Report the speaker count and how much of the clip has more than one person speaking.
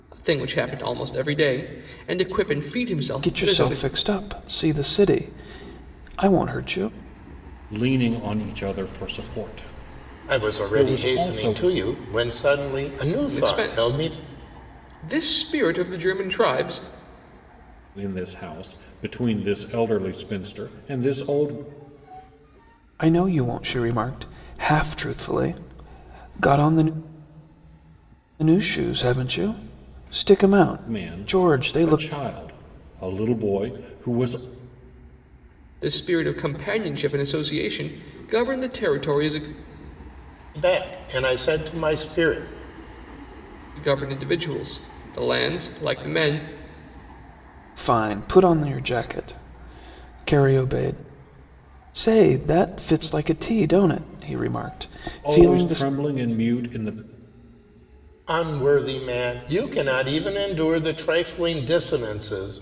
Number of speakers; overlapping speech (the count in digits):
4, about 7%